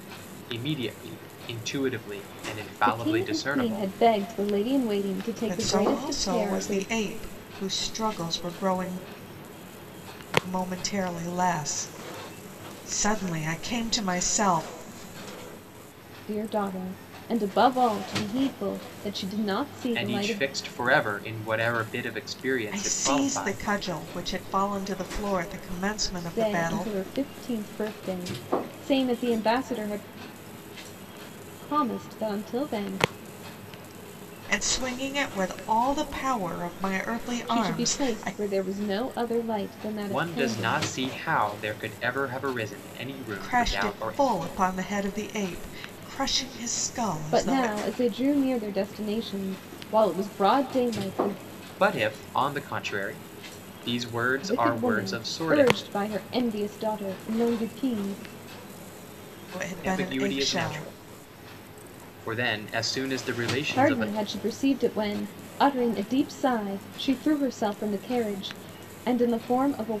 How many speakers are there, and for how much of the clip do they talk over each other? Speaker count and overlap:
three, about 16%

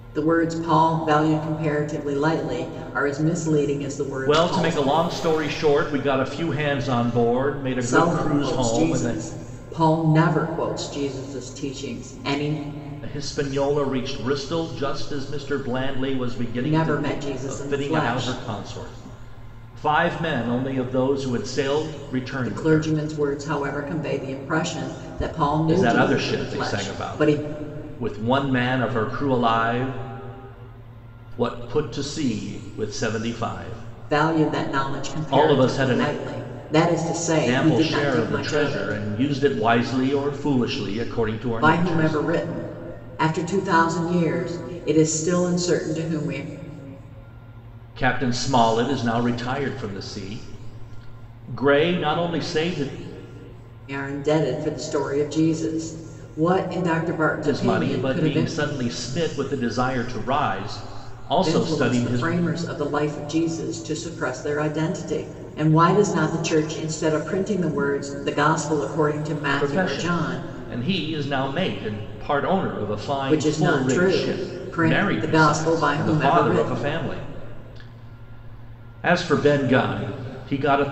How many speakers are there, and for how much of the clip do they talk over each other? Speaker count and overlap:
two, about 21%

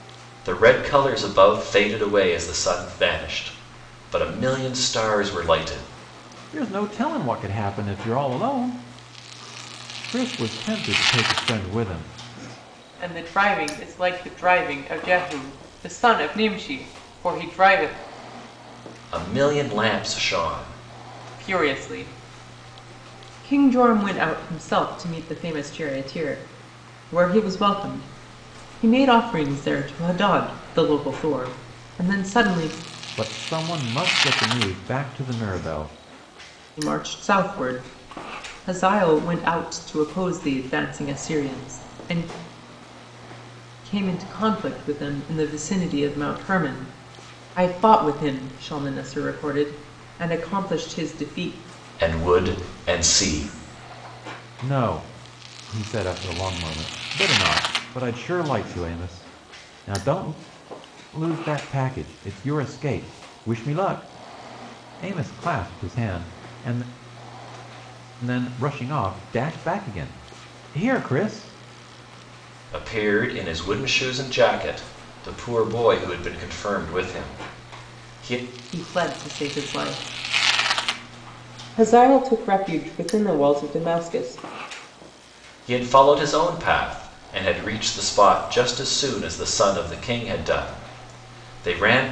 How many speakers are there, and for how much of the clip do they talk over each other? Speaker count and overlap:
three, no overlap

